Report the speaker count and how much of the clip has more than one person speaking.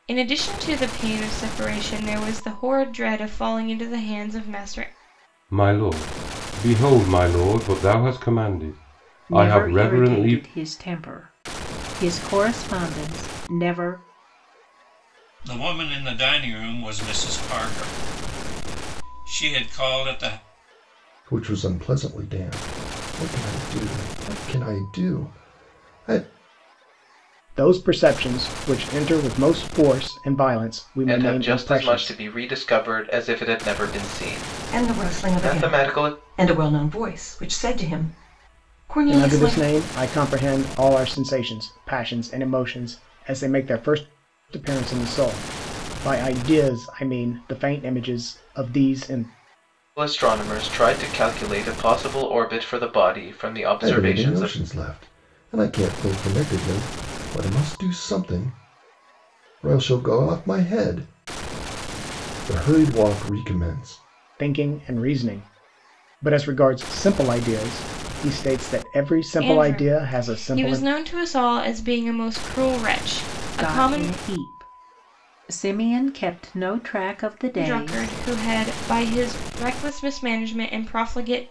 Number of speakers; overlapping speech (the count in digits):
8, about 9%